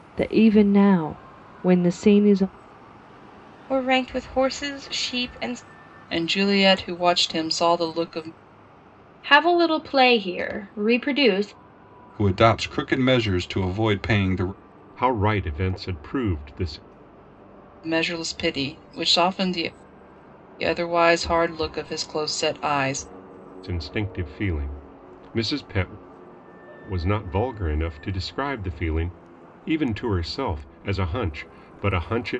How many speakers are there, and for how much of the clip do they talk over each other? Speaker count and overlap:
six, no overlap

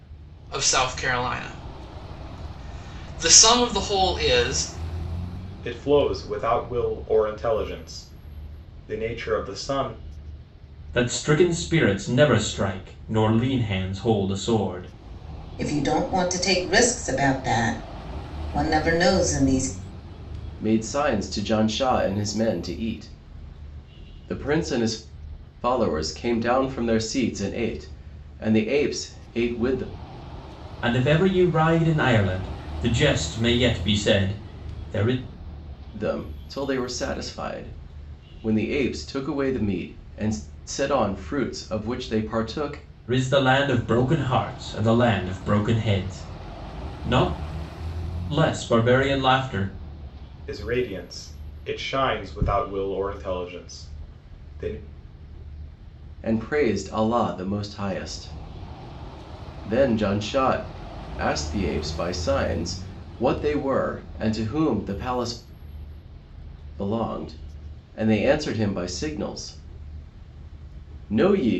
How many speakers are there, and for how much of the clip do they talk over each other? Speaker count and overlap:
five, no overlap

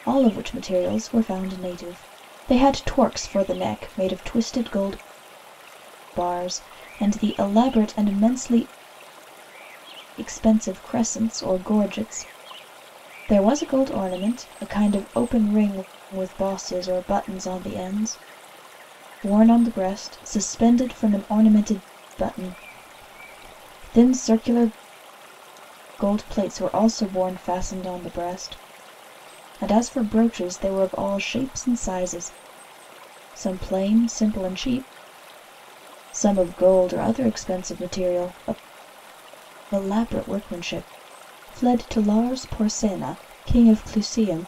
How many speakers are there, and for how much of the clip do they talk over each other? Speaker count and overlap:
one, no overlap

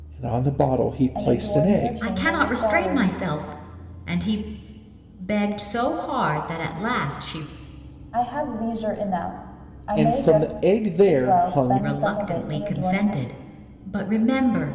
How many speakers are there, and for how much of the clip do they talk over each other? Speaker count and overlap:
three, about 33%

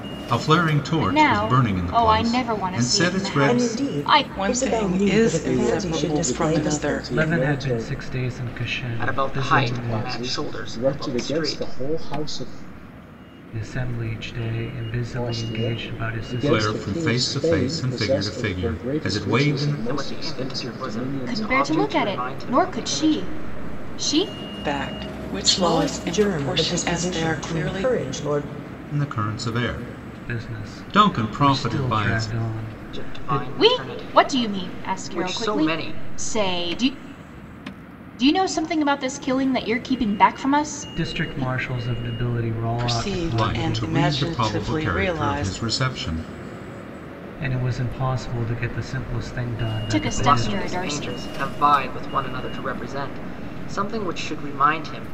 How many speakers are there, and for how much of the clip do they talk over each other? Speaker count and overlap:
seven, about 55%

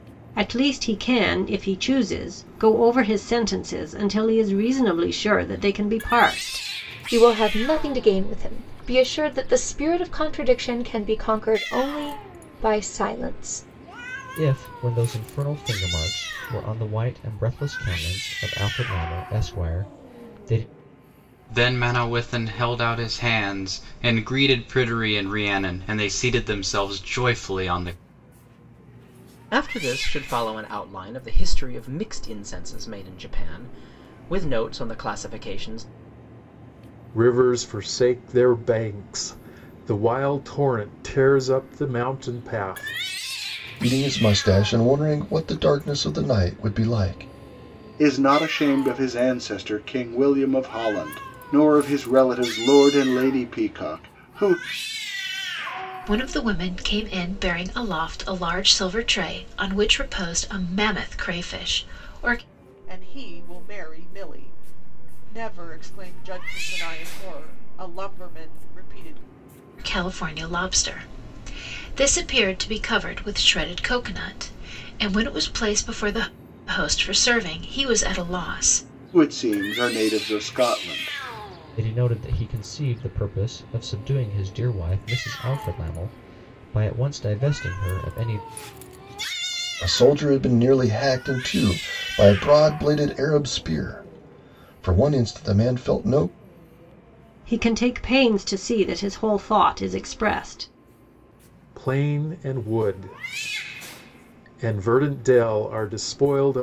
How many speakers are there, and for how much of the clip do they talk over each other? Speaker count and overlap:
ten, no overlap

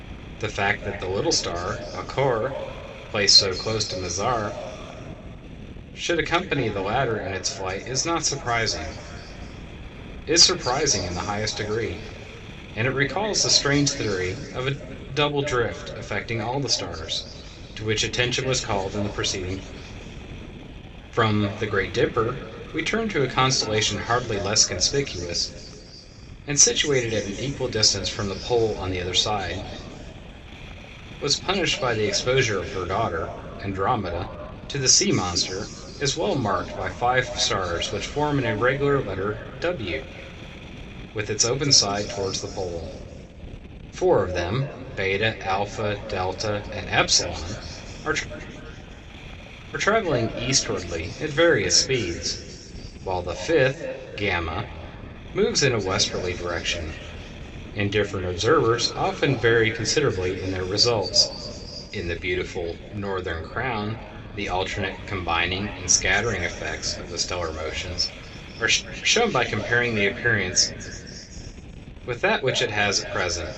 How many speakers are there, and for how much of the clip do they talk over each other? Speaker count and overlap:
one, no overlap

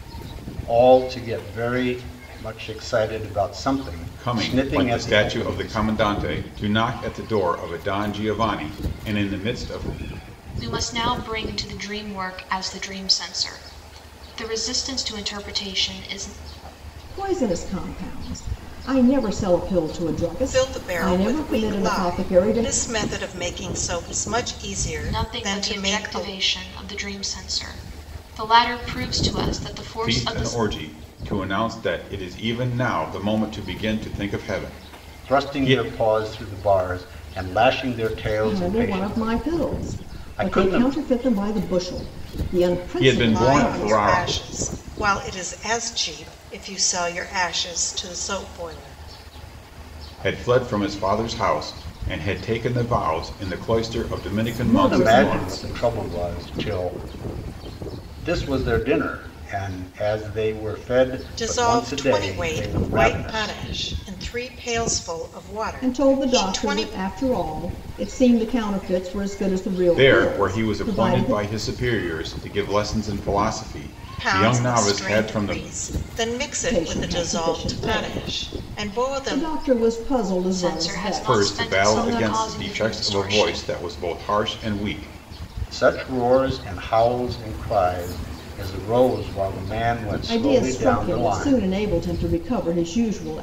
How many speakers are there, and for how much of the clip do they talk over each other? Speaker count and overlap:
five, about 27%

